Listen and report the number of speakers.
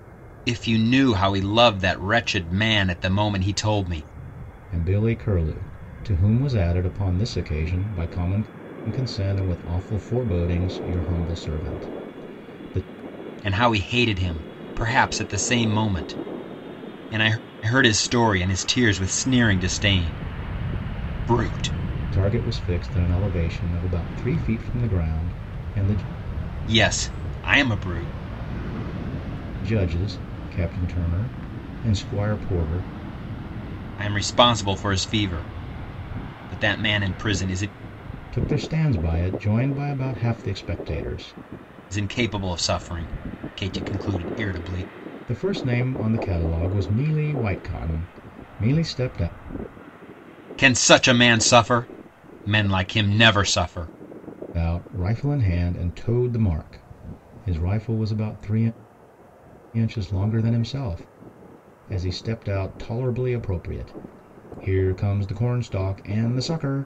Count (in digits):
2